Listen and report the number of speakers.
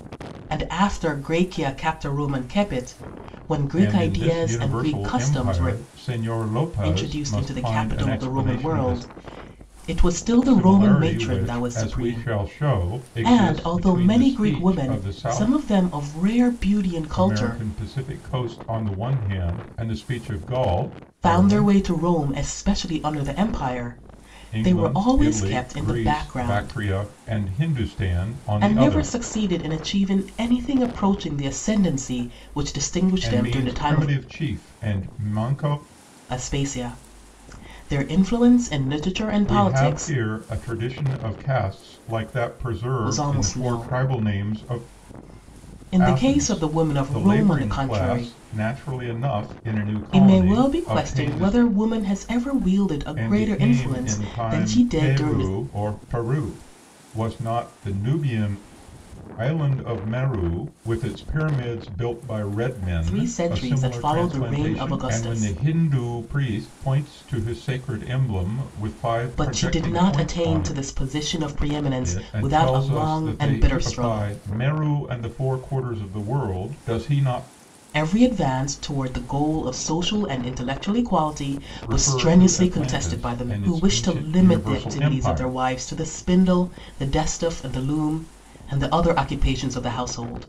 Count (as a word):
two